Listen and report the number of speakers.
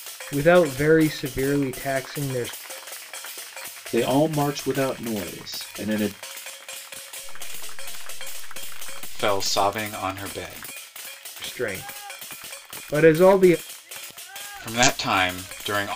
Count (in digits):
4